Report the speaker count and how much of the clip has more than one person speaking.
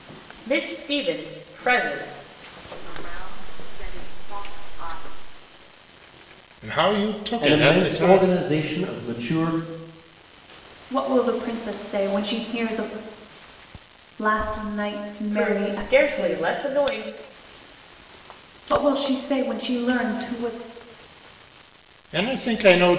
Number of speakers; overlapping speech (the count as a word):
five, about 10%